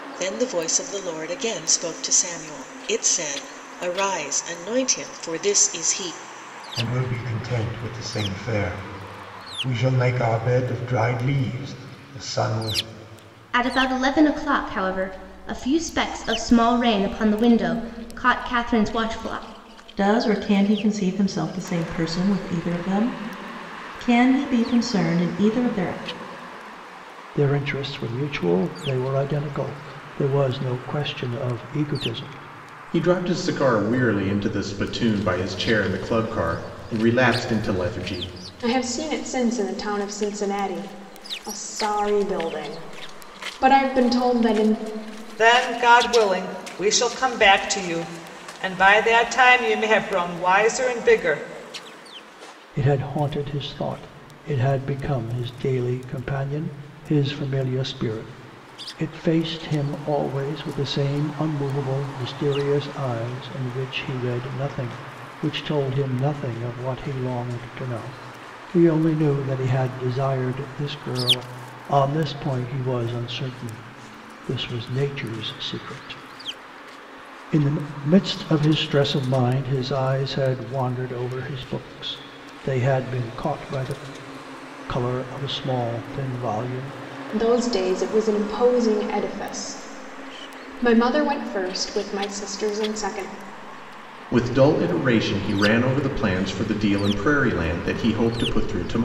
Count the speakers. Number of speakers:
8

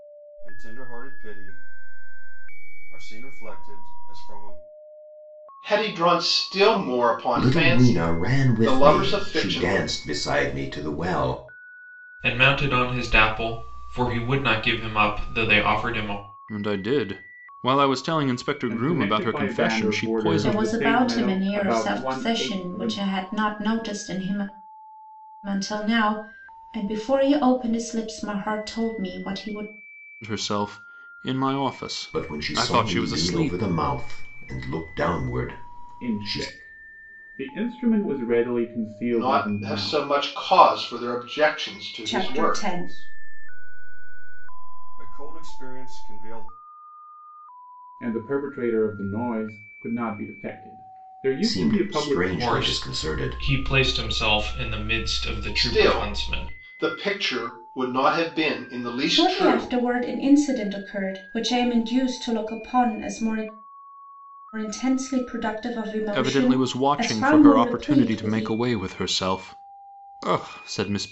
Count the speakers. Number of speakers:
7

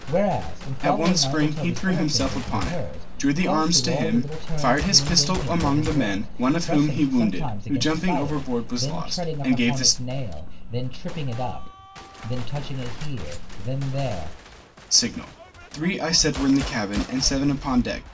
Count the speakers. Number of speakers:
2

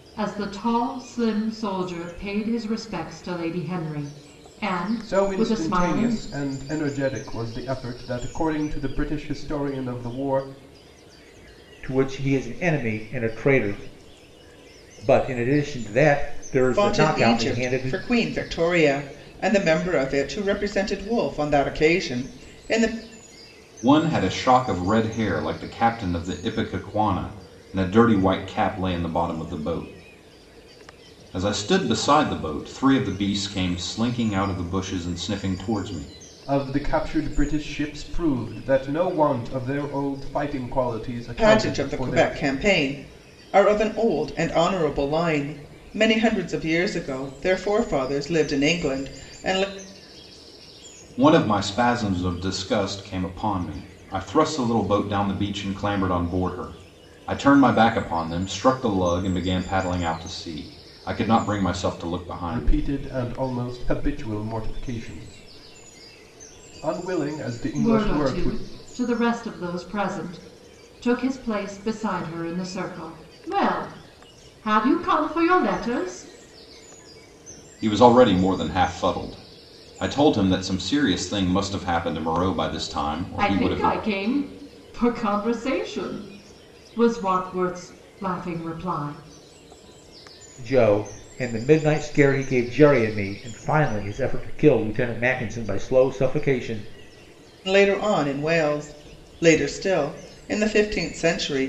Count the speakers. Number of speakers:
5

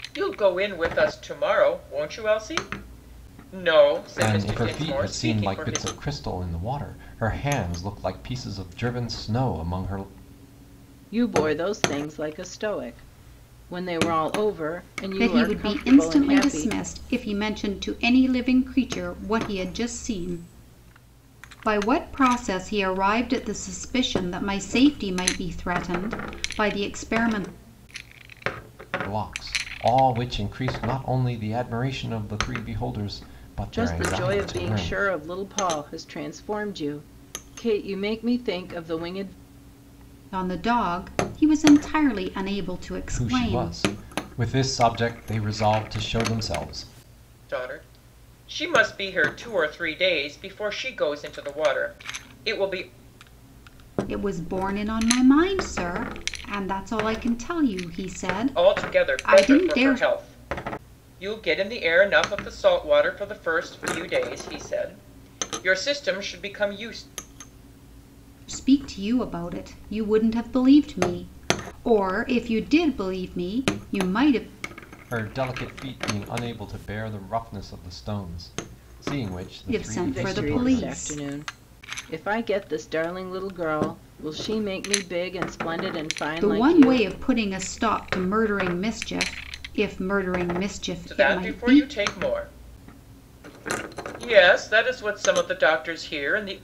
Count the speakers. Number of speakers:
4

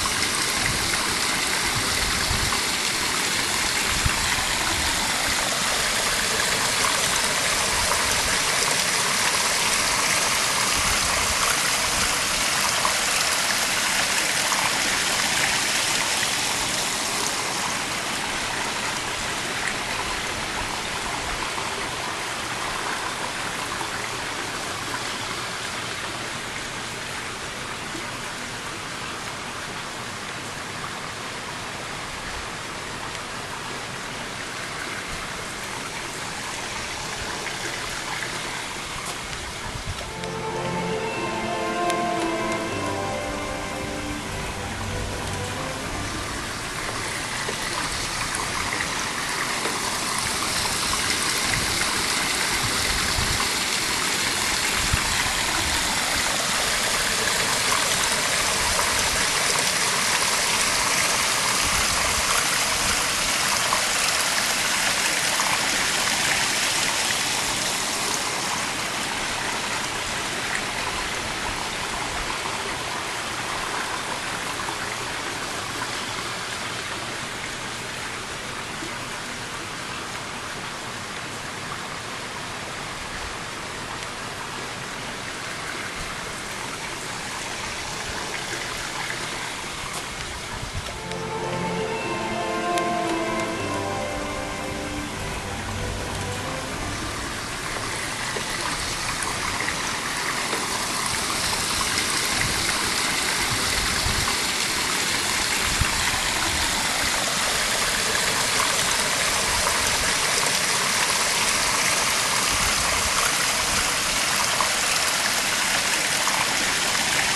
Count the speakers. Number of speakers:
0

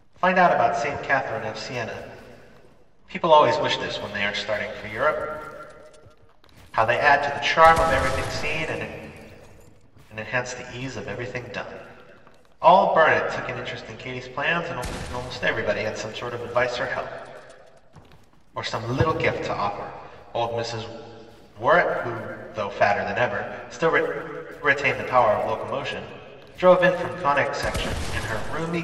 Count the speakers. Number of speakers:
1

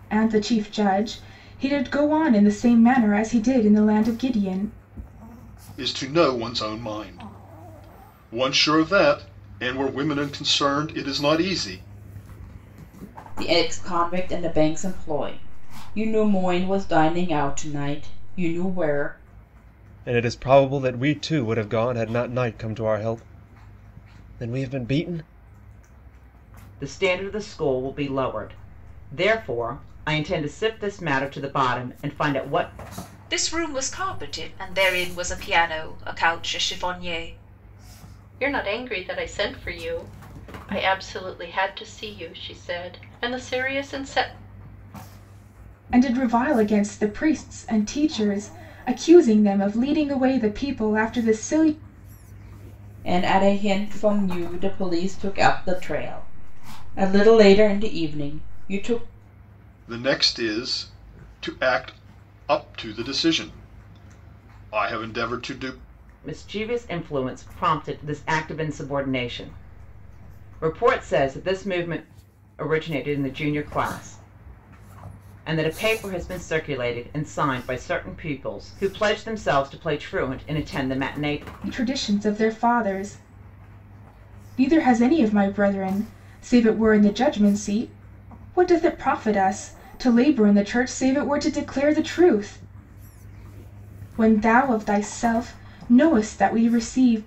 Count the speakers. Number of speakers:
7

